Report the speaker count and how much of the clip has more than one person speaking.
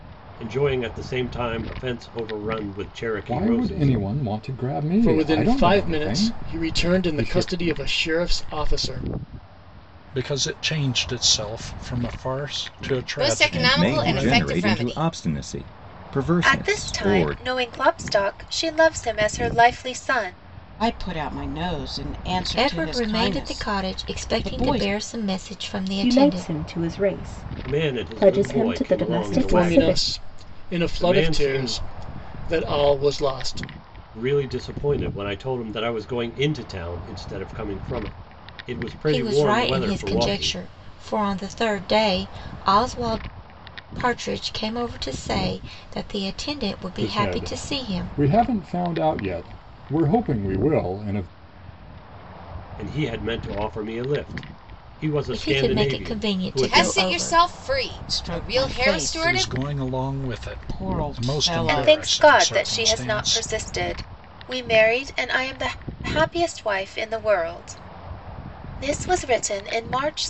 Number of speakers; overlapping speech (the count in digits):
10, about 34%